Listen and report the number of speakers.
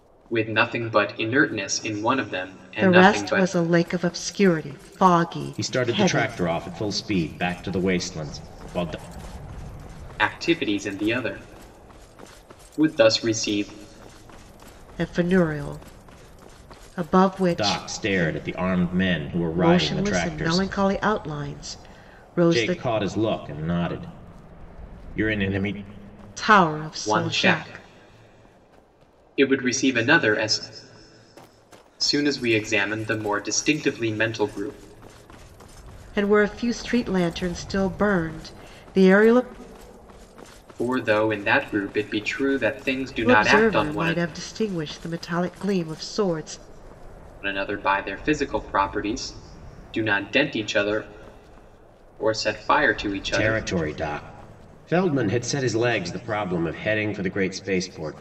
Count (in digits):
3